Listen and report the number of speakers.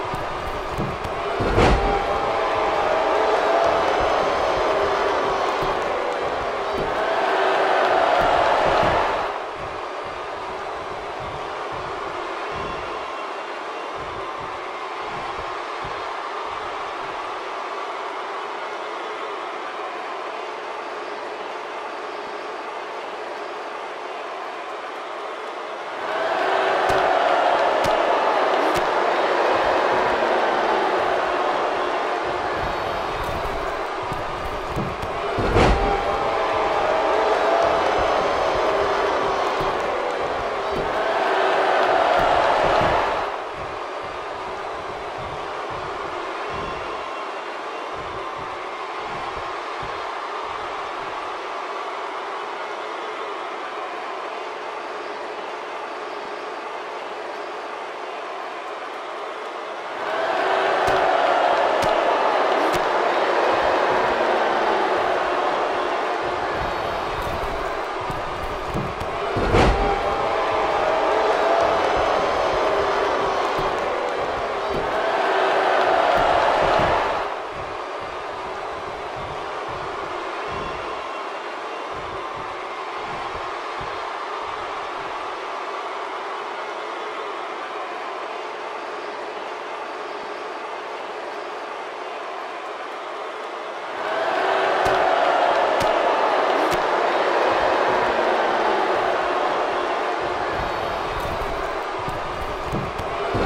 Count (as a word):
zero